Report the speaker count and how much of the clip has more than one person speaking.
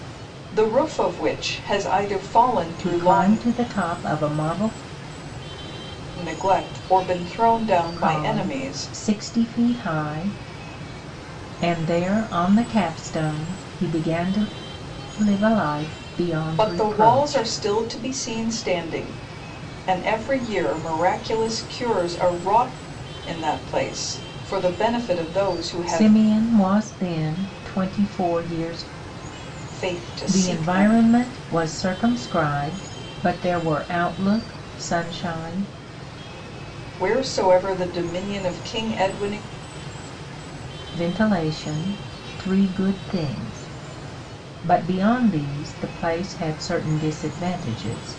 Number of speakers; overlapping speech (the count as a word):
two, about 8%